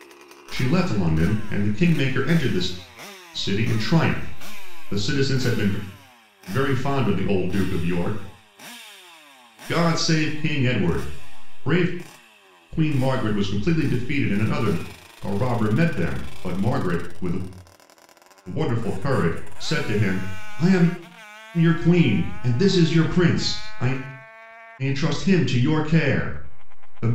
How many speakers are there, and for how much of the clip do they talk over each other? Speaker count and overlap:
1, no overlap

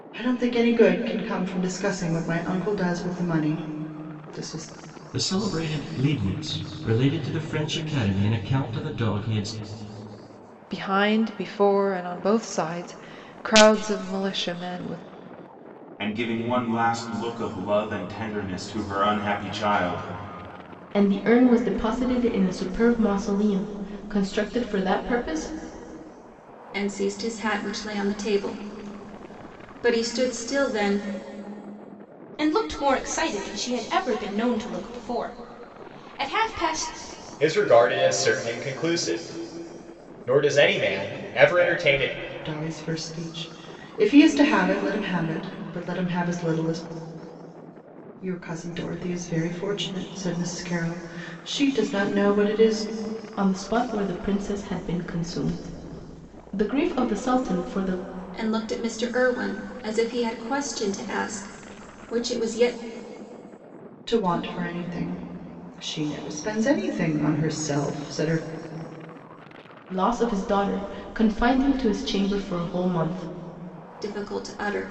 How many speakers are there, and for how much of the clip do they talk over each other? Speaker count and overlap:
8, no overlap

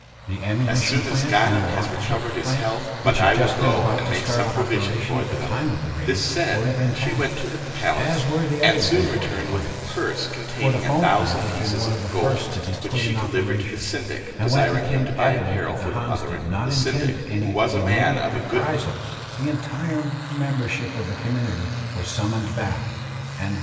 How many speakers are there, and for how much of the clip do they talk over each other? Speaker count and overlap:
2, about 74%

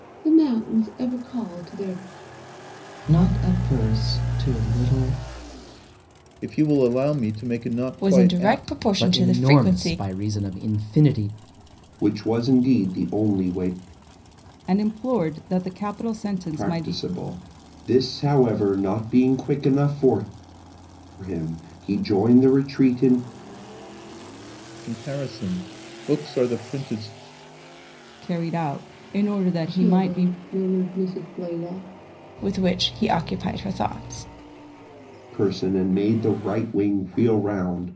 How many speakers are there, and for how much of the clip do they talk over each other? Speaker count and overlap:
7, about 8%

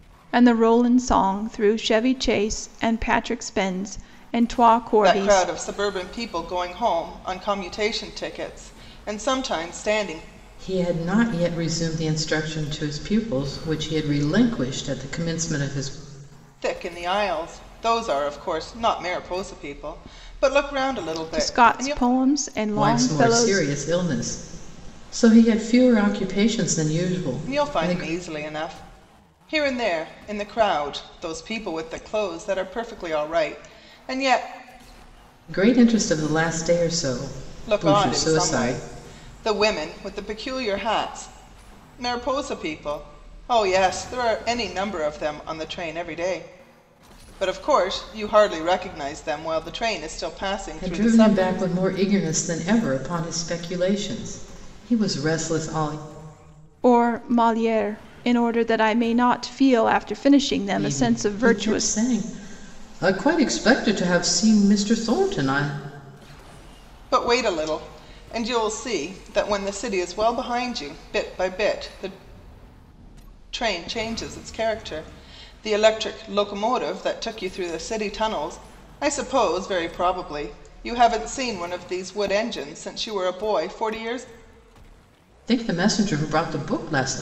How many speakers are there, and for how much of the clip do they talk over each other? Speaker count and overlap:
3, about 7%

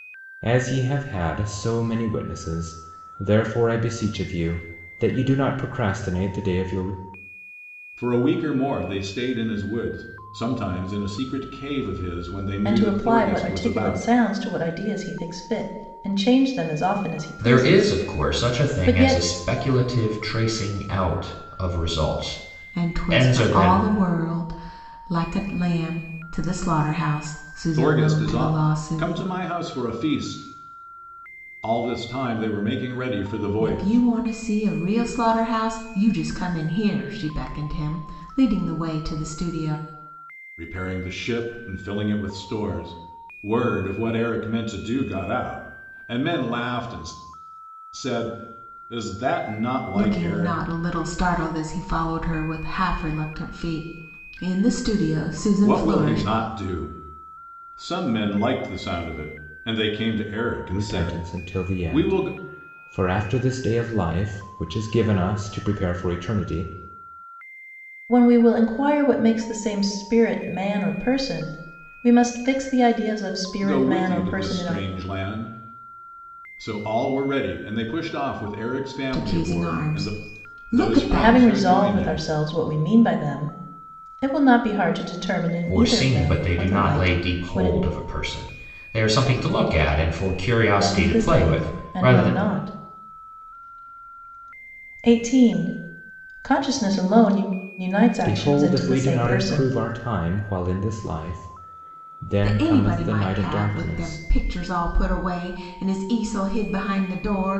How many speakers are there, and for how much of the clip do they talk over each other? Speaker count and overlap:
5, about 19%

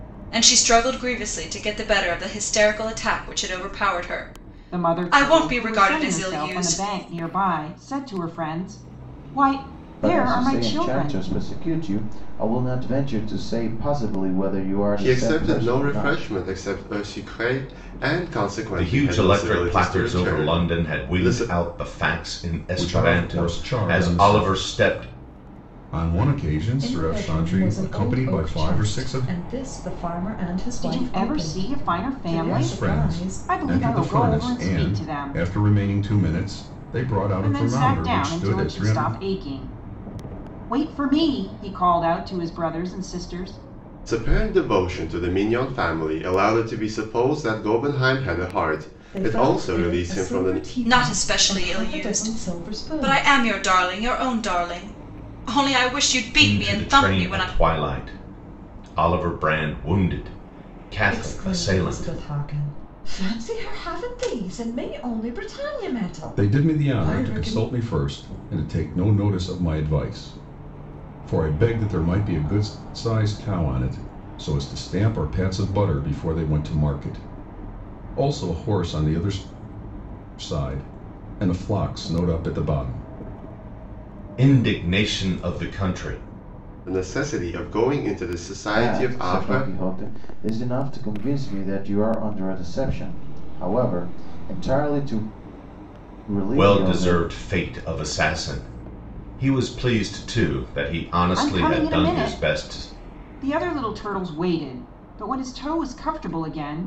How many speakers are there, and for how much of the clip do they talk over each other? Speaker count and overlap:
7, about 28%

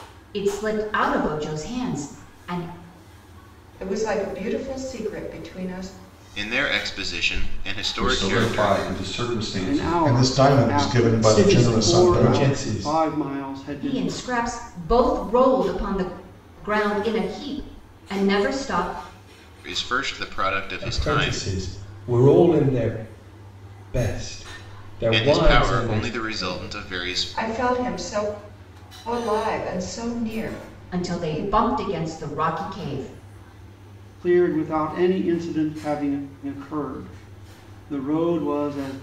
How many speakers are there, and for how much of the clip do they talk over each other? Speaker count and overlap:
7, about 20%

